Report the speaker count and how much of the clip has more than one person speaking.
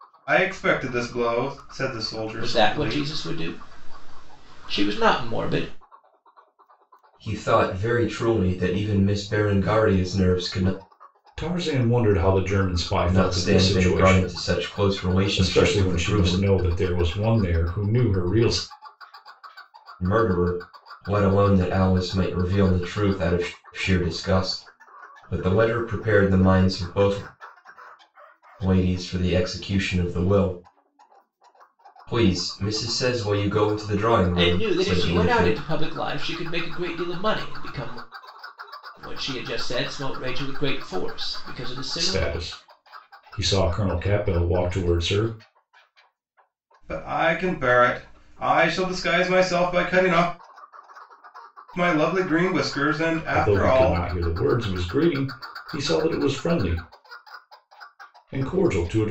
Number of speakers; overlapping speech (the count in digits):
4, about 9%